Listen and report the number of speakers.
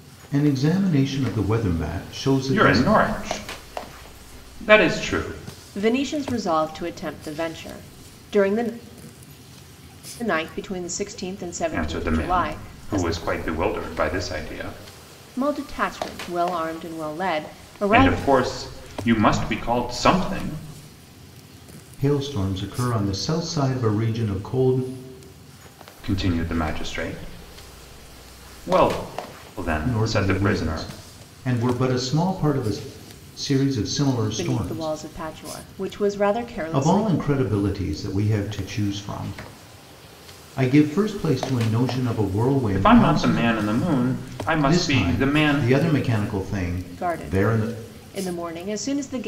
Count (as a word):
three